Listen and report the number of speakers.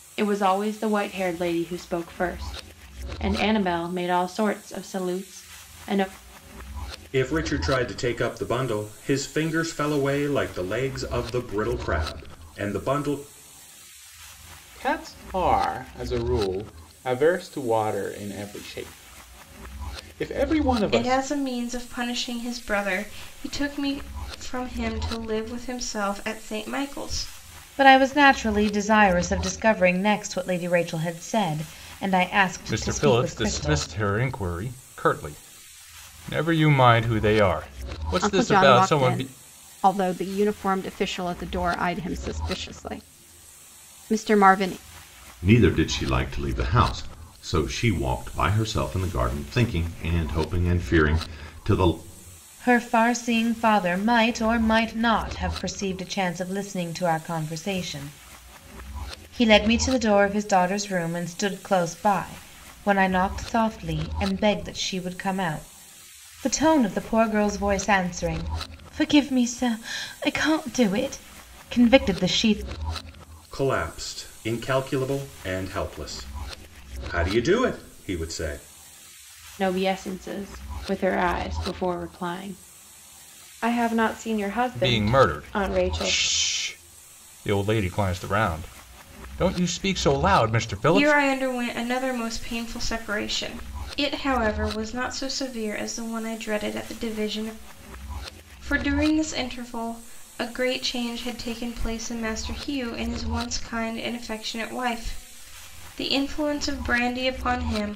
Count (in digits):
8